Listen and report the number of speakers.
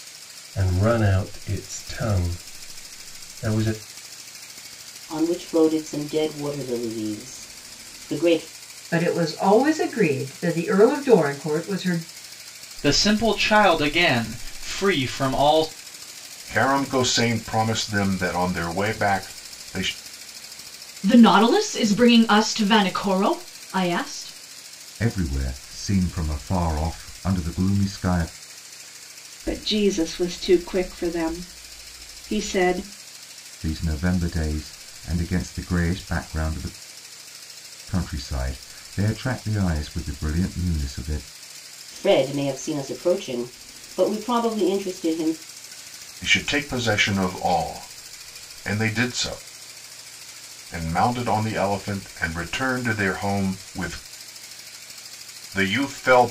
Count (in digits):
8